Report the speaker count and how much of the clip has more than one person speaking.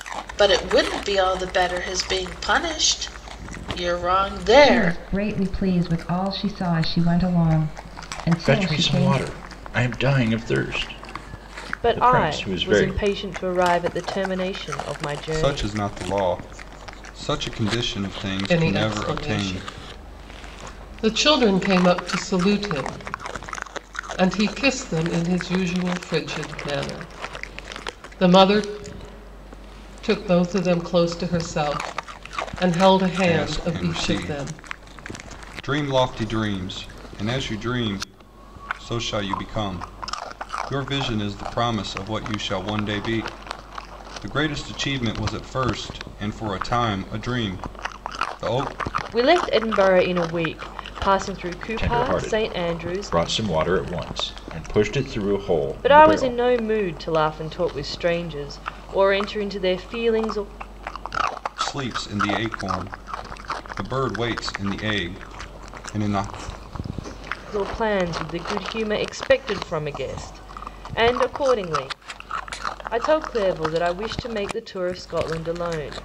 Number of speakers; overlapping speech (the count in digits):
6, about 10%